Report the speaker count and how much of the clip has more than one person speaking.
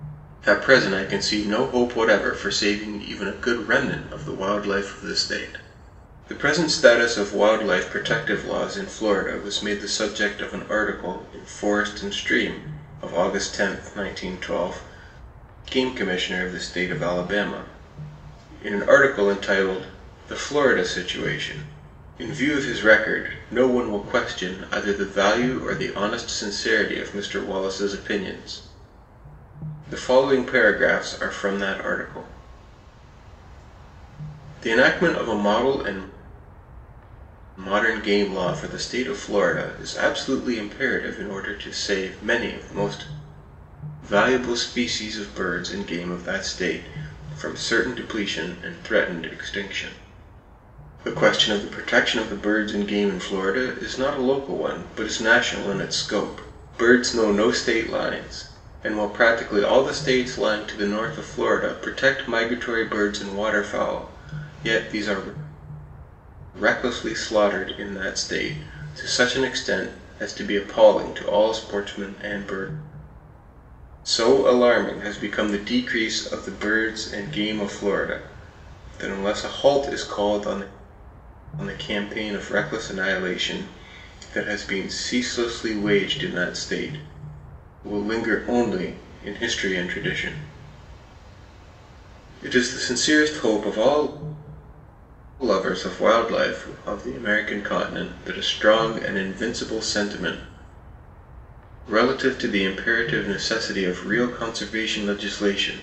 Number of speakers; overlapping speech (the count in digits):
1, no overlap